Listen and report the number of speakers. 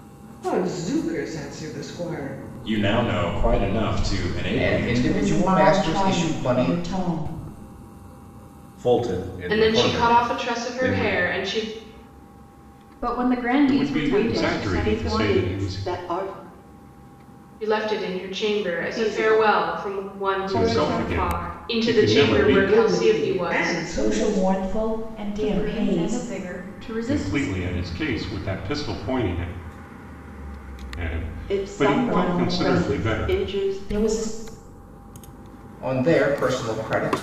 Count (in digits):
9